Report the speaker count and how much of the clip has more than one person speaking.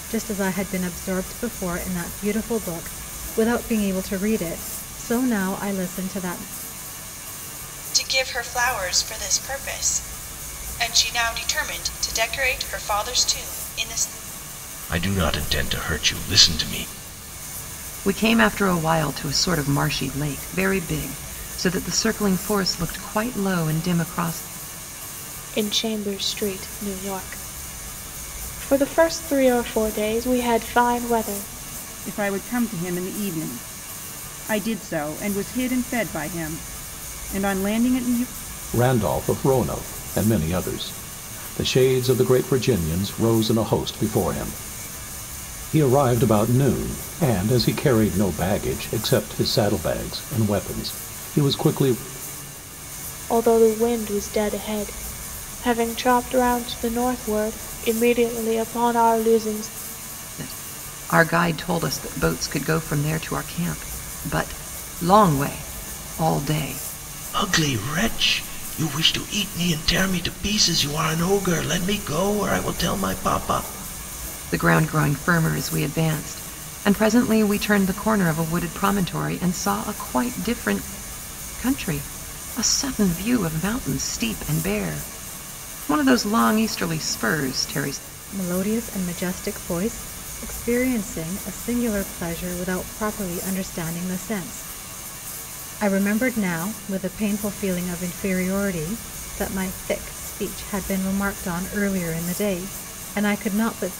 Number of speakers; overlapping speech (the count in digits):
7, no overlap